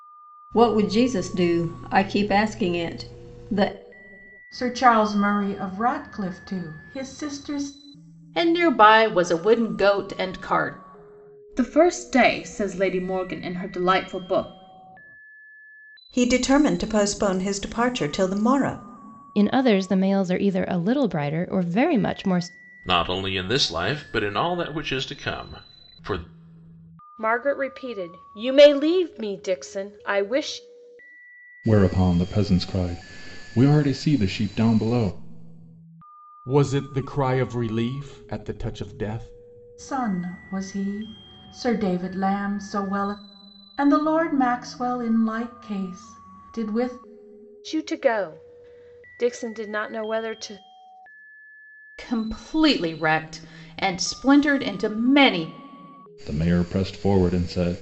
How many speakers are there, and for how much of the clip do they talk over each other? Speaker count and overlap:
ten, no overlap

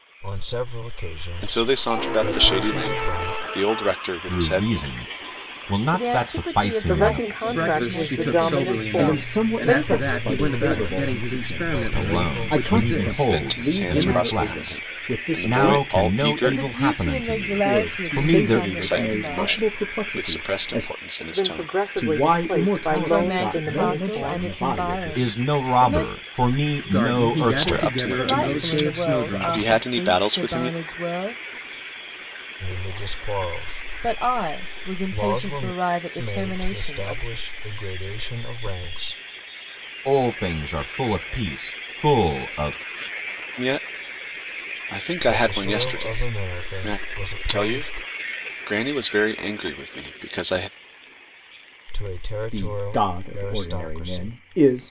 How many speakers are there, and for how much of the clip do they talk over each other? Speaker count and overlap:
seven, about 62%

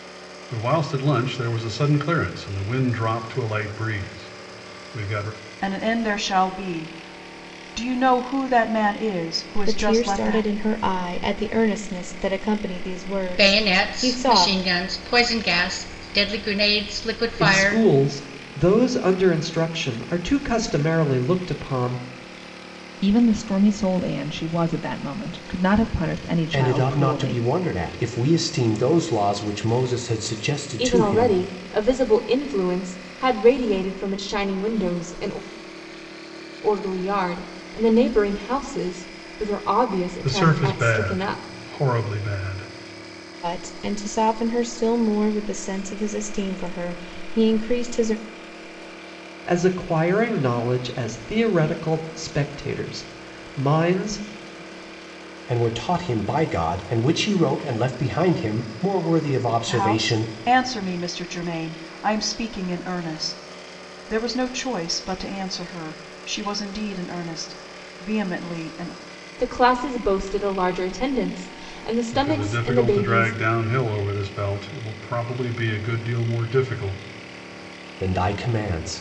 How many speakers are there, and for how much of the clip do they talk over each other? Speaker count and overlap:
eight, about 9%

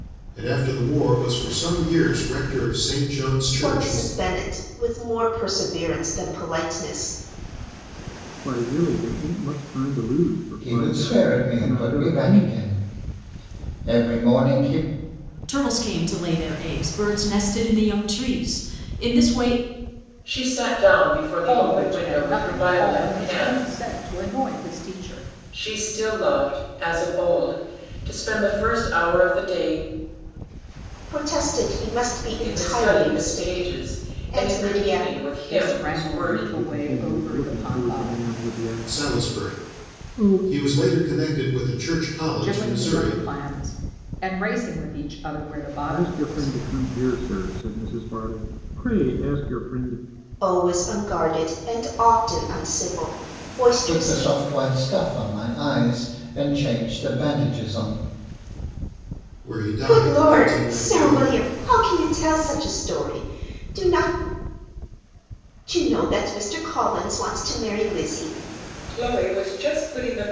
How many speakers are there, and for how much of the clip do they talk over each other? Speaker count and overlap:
seven, about 22%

